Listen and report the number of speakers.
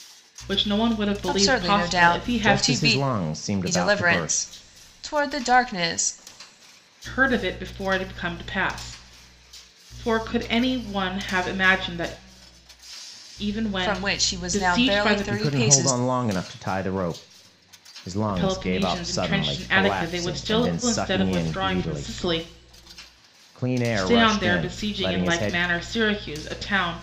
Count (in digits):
3